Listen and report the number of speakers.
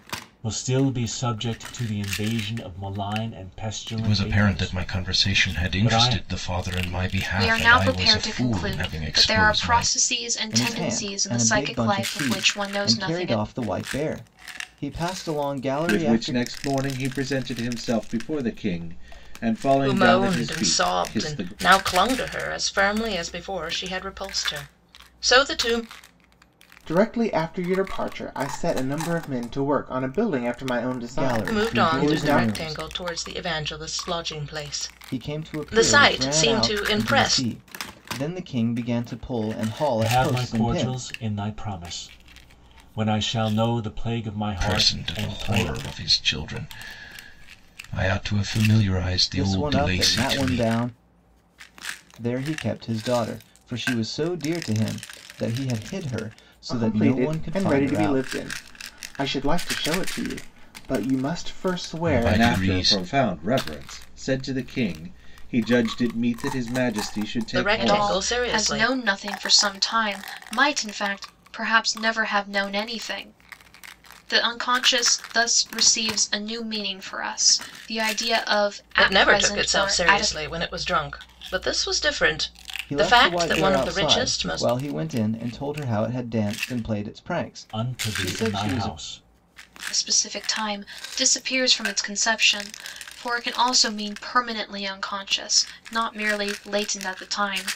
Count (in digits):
7